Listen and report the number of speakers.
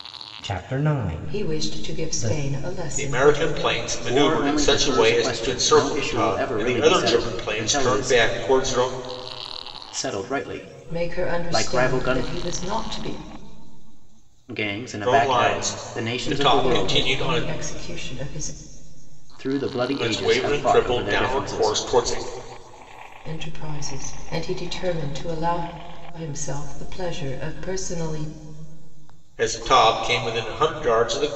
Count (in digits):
4